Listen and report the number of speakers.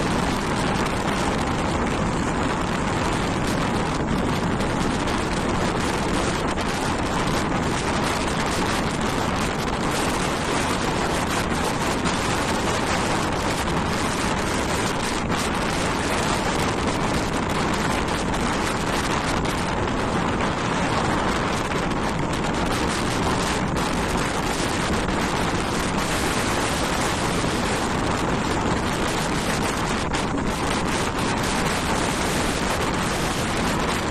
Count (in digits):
0